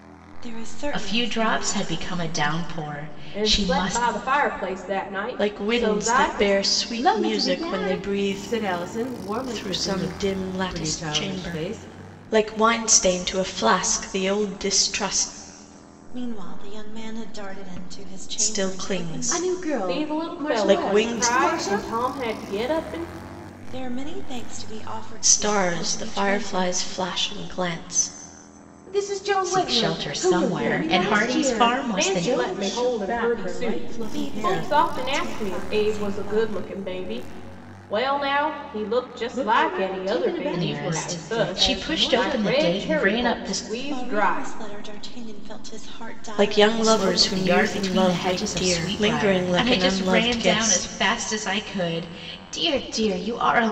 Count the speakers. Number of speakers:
5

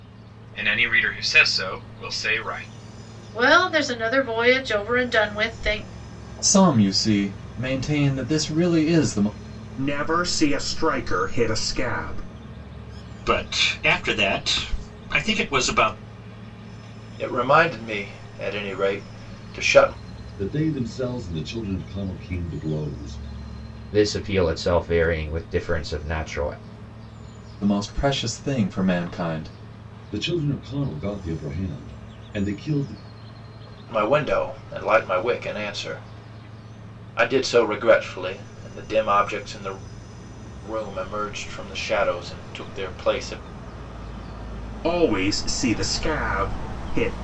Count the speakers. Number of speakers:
8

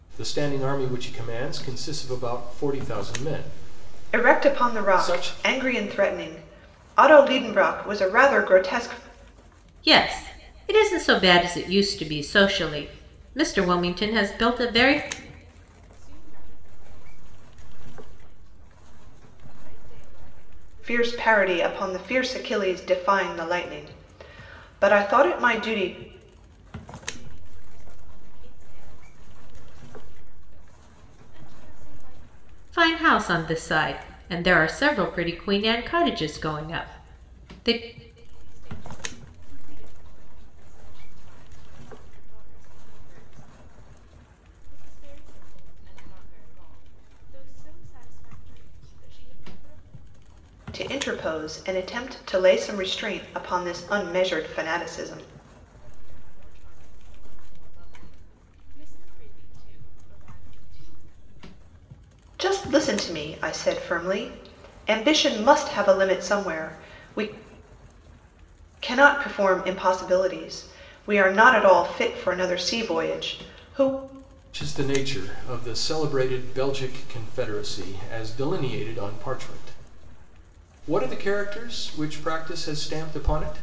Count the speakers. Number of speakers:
4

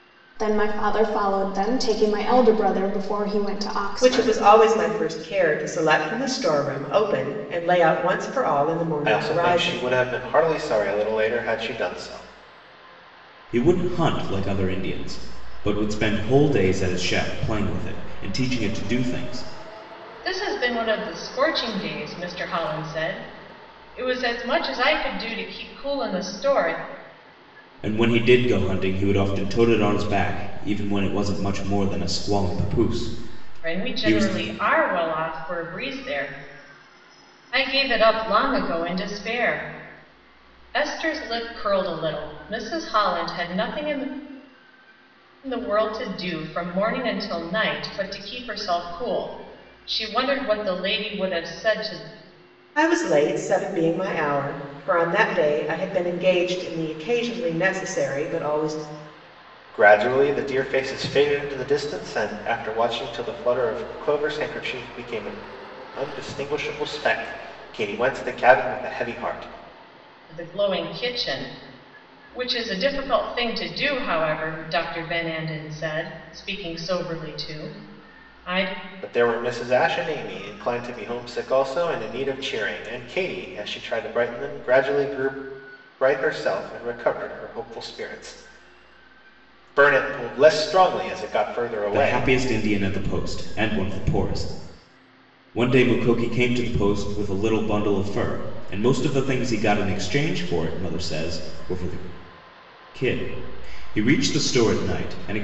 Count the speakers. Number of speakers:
5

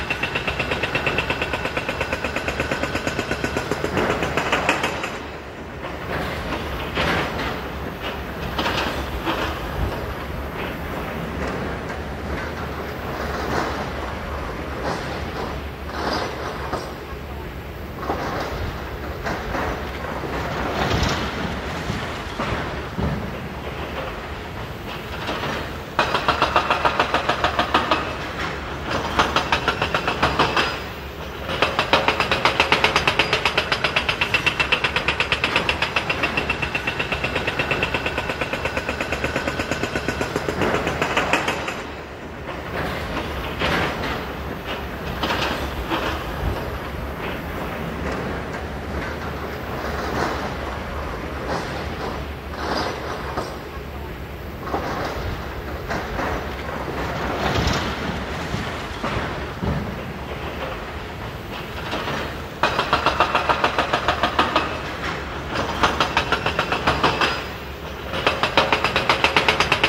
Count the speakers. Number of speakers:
0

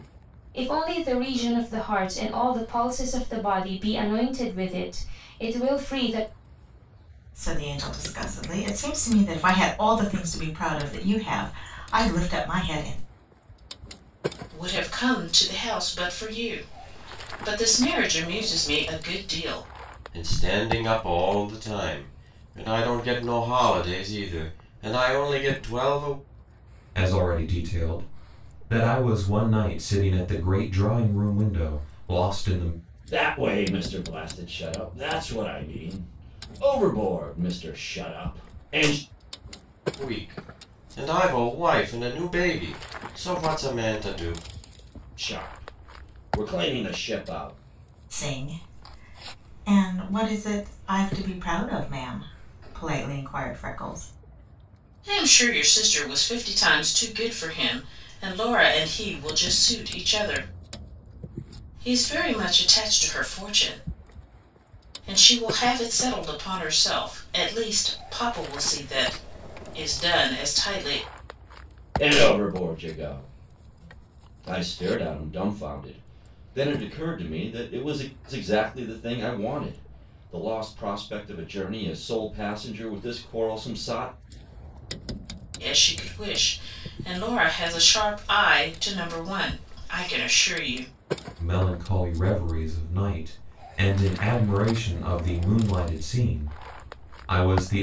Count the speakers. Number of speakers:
6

